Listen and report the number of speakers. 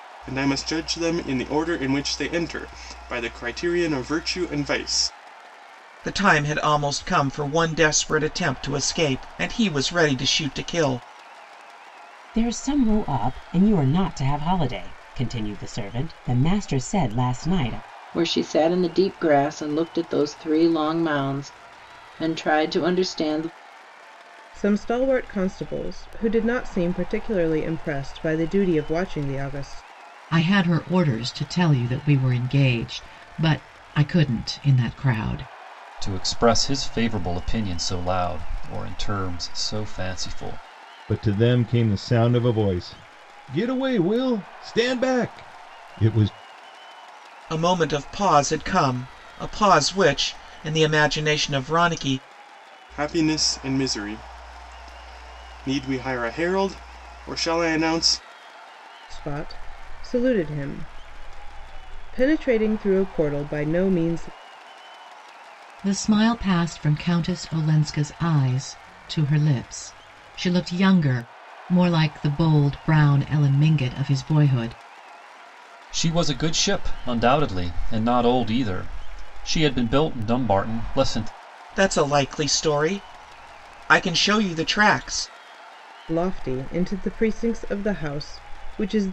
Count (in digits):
8